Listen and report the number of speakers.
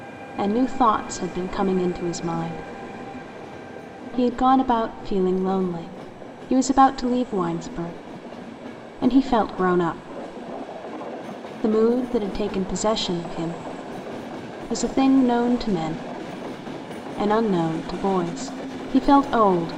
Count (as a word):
one